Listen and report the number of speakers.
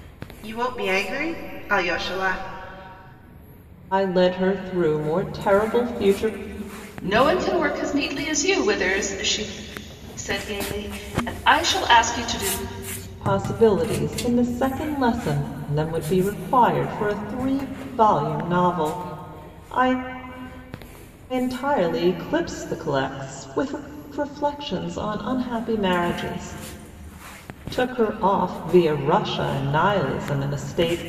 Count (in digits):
3